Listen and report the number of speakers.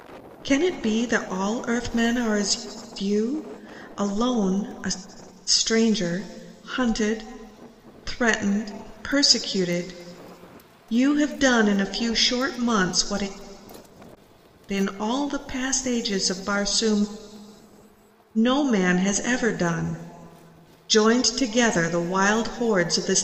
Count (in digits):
1